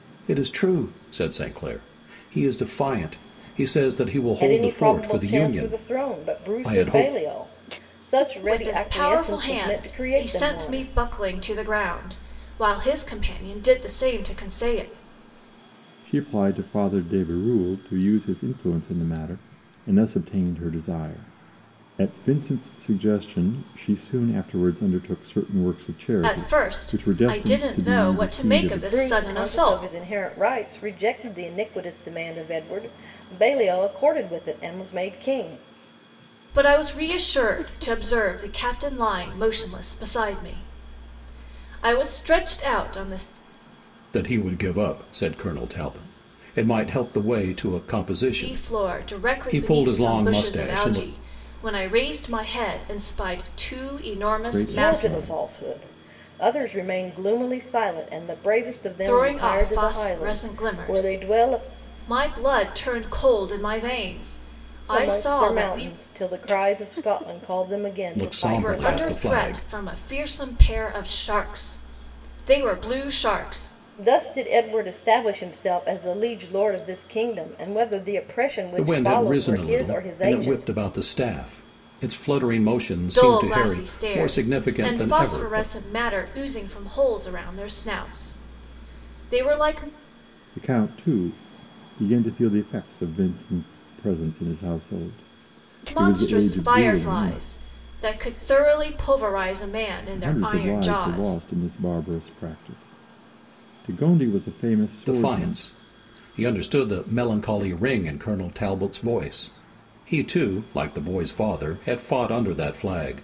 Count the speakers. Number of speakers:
four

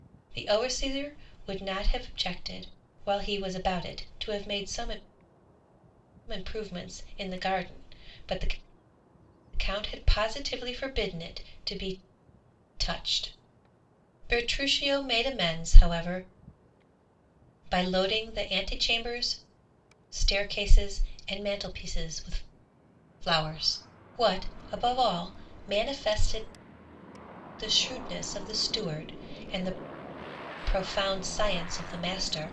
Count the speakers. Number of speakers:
one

